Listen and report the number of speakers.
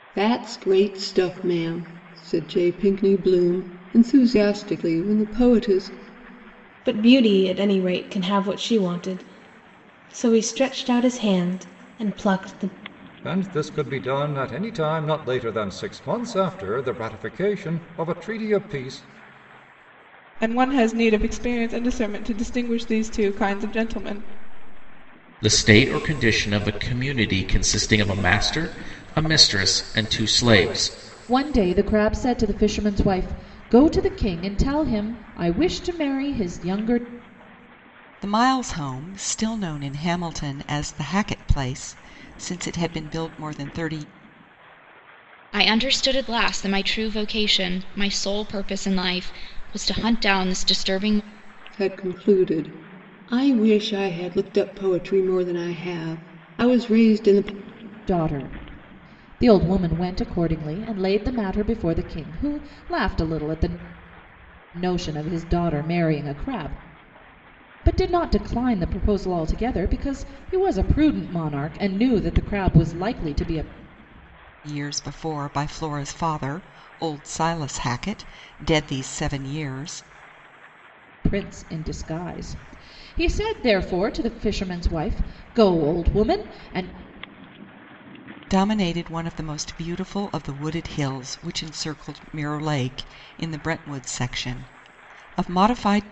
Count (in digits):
8